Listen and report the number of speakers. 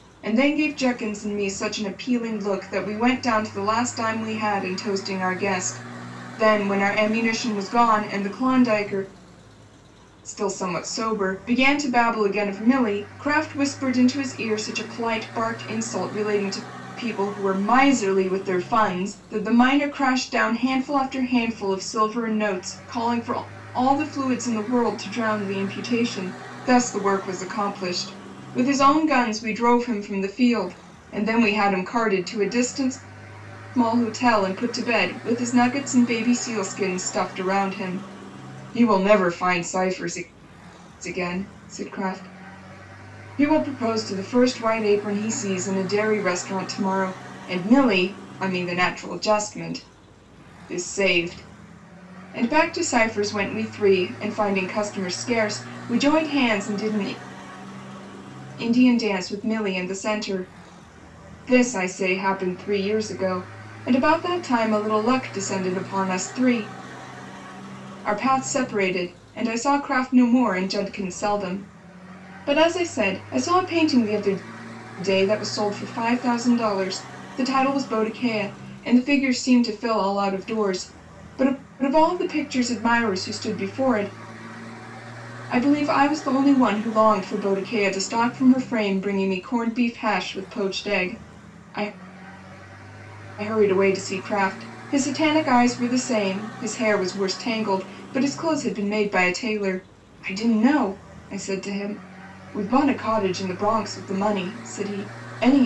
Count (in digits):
1